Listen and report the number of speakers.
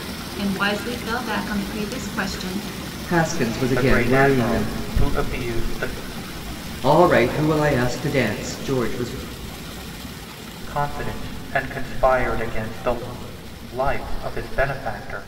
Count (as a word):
three